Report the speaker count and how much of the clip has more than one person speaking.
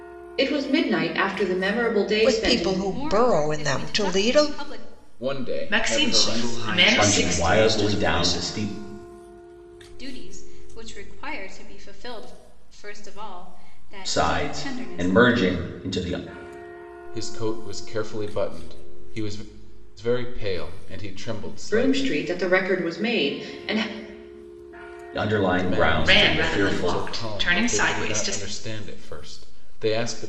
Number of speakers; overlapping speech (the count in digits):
7, about 32%